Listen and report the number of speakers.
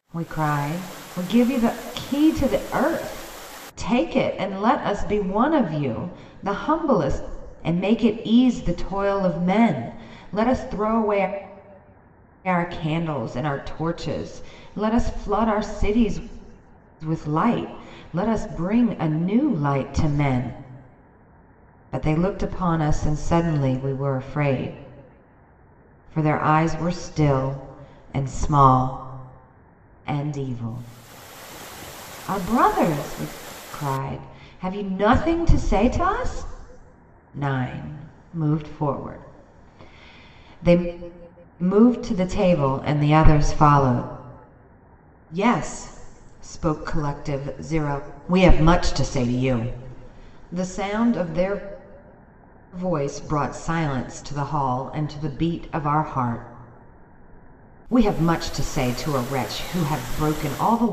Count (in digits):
1